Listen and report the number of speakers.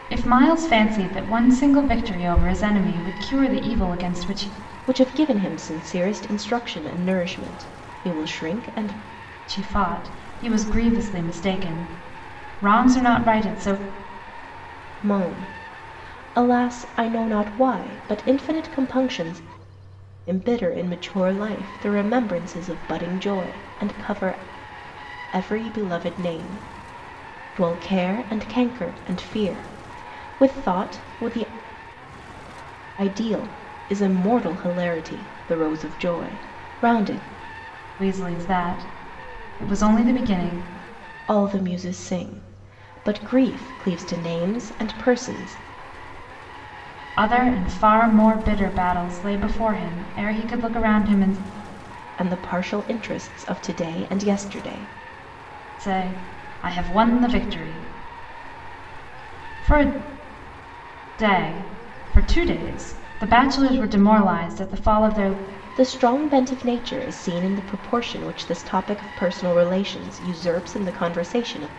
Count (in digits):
2